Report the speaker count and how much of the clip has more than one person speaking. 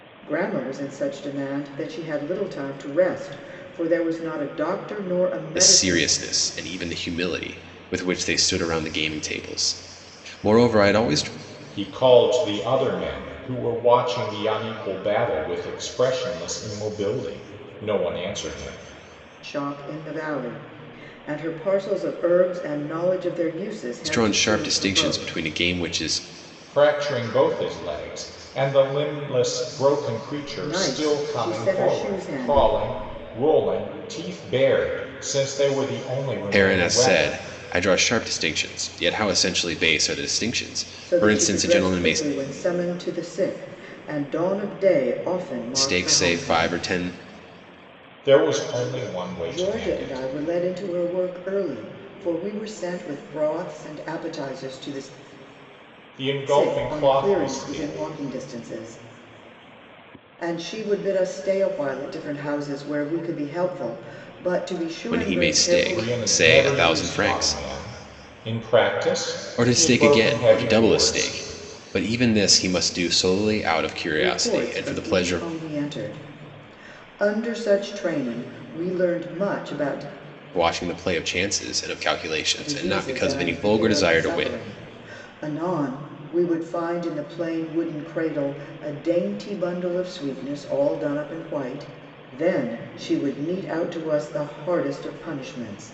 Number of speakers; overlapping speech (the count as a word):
three, about 18%